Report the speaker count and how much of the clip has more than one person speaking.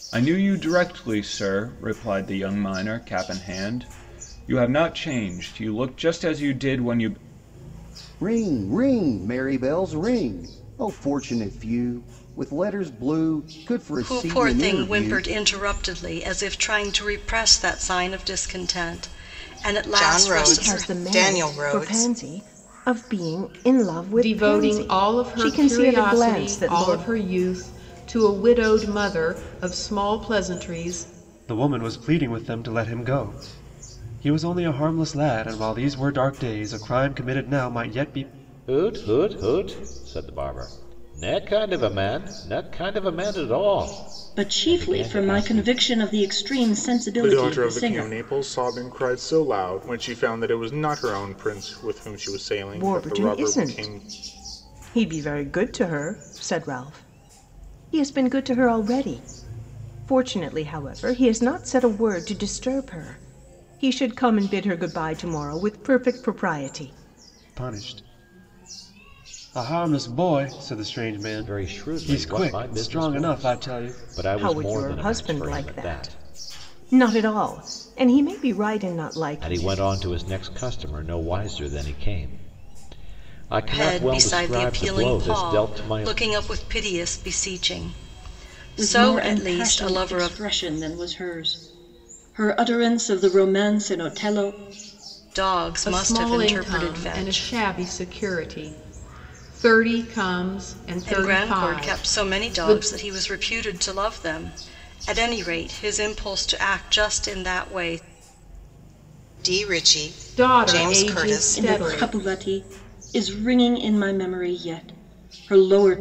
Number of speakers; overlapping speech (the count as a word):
ten, about 21%